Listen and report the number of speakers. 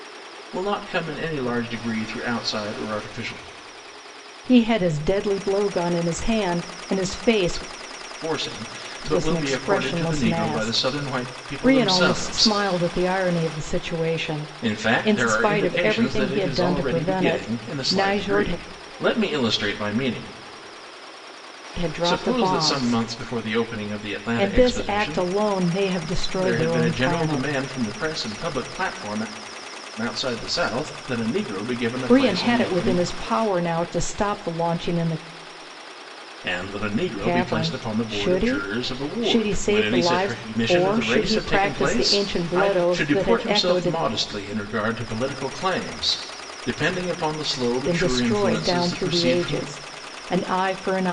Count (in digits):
2